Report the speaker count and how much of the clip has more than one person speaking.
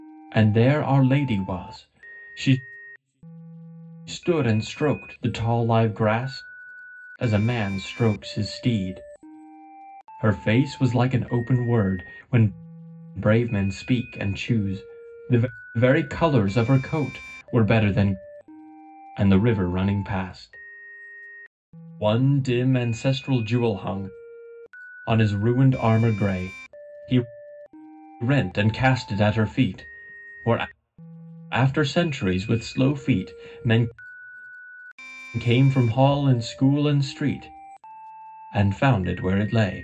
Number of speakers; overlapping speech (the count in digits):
1, no overlap